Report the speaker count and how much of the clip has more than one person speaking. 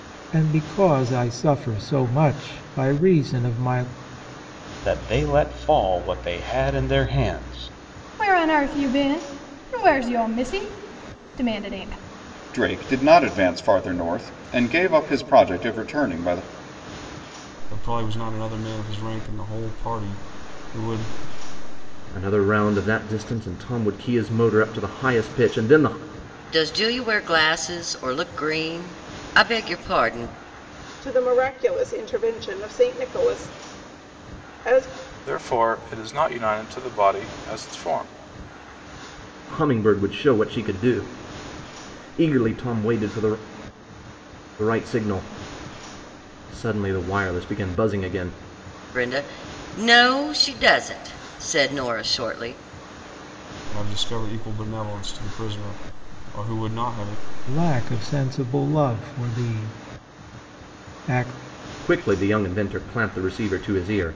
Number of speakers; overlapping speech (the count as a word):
nine, no overlap